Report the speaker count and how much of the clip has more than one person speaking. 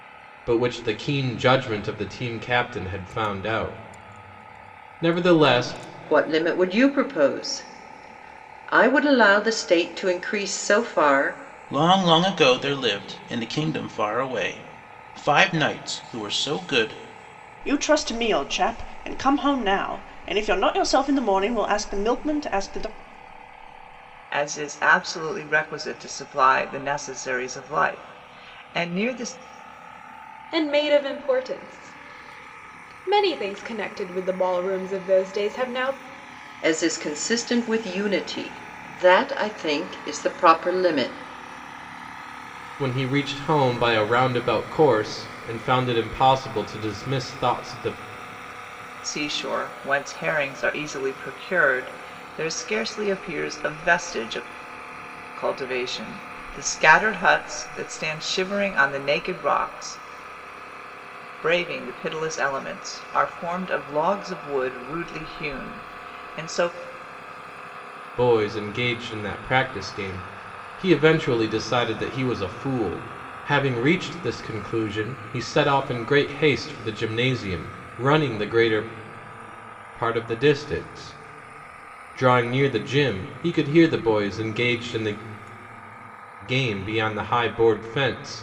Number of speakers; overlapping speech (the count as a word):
six, no overlap